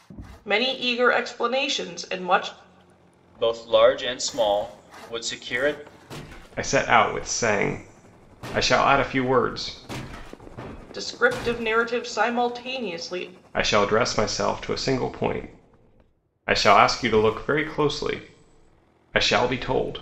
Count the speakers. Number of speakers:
3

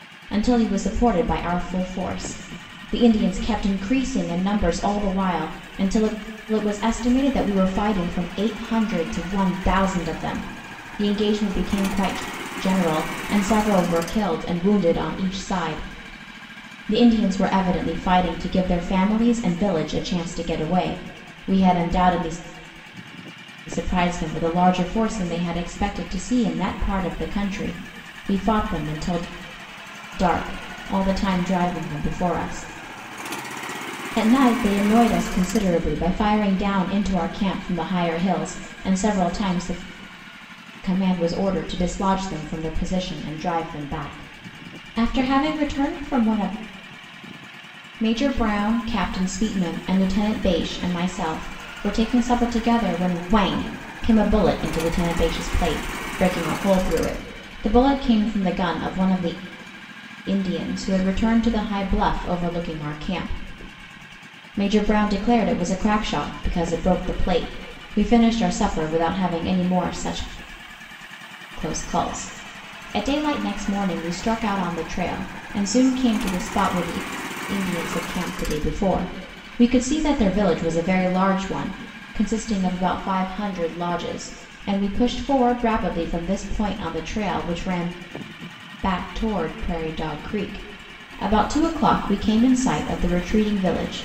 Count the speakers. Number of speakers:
1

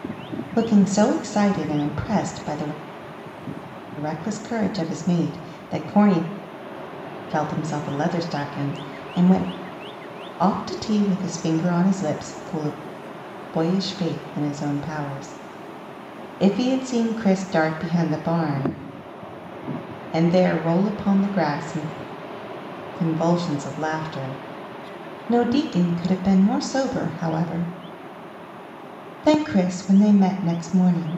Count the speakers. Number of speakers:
1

